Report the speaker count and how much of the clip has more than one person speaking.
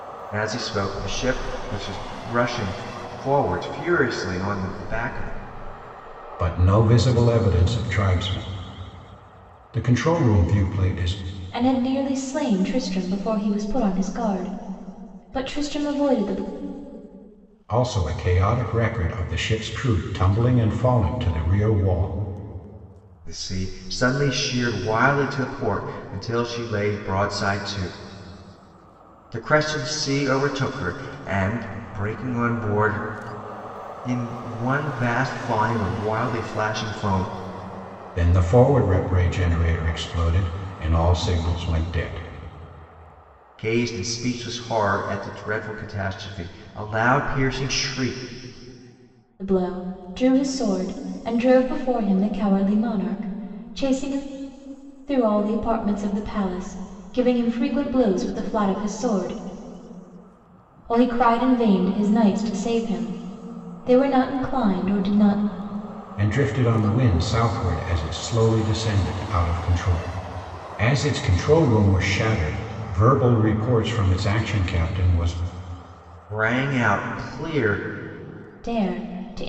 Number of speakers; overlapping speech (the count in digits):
3, no overlap